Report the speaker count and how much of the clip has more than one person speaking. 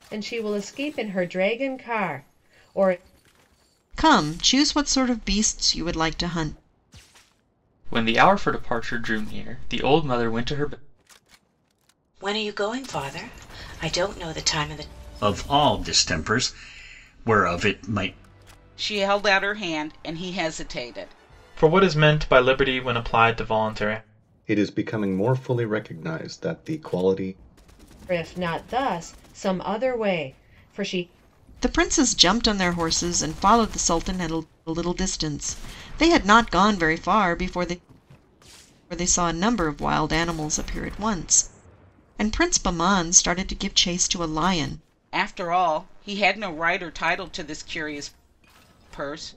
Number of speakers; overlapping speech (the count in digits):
8, no overlap